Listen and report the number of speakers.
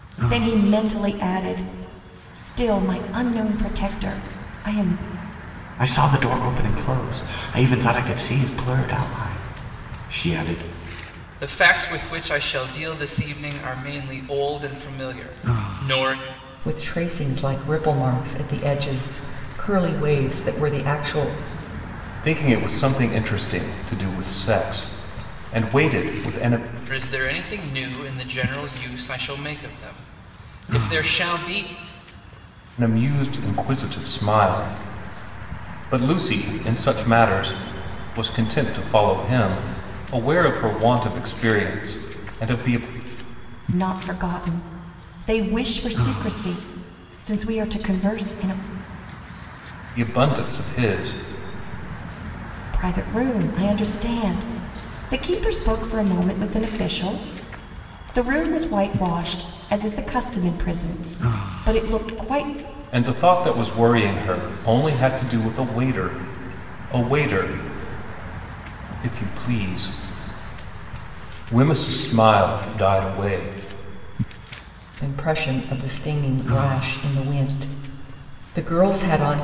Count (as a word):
five